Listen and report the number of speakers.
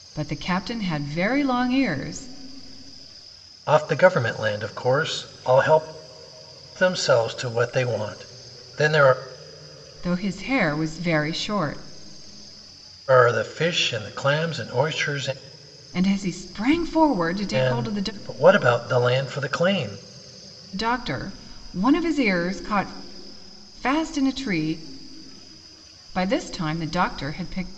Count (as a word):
two